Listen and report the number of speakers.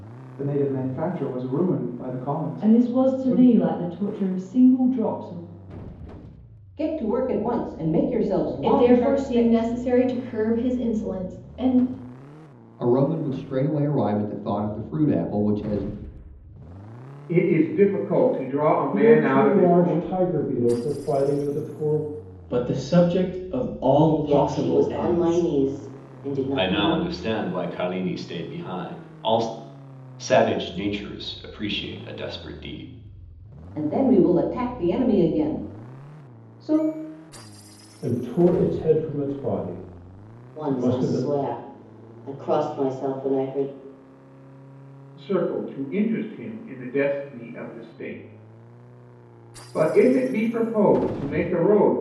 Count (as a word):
ten